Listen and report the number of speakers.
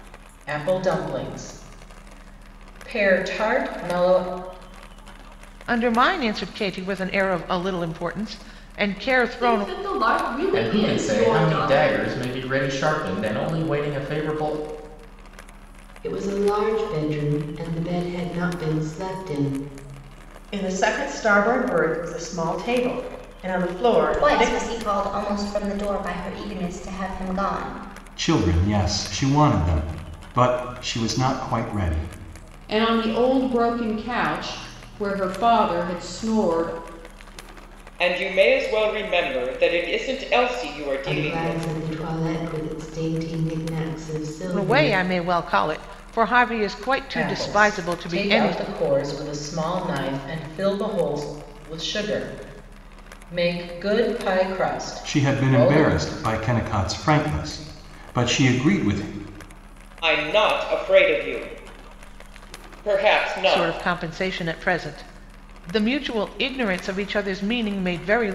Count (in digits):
10